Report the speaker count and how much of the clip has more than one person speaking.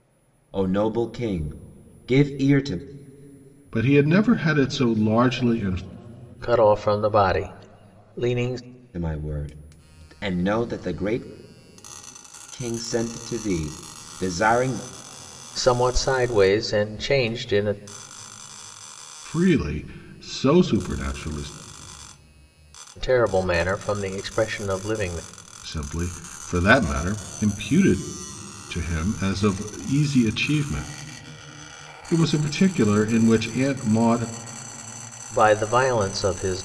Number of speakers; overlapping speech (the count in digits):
3, no overlap